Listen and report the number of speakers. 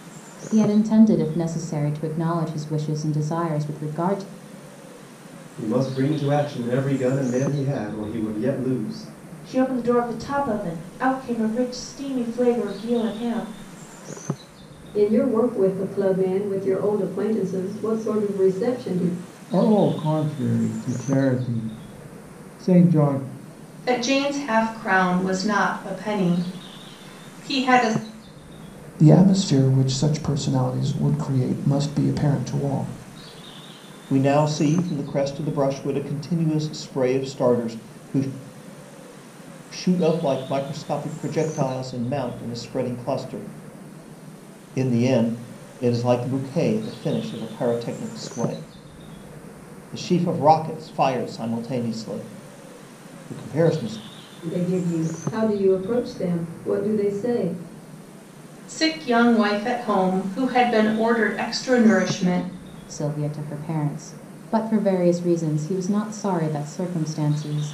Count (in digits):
8